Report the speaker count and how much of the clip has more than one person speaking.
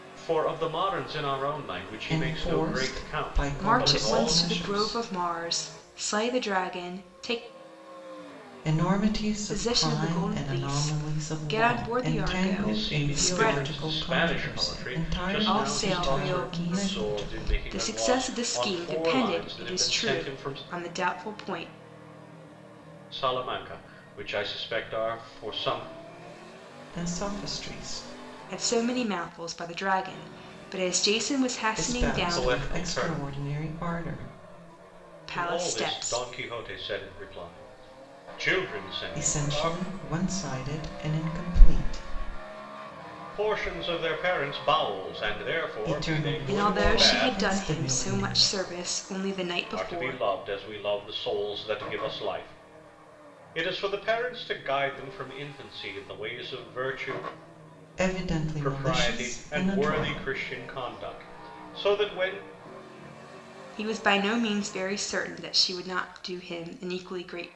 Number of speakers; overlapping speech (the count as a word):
three, about 34%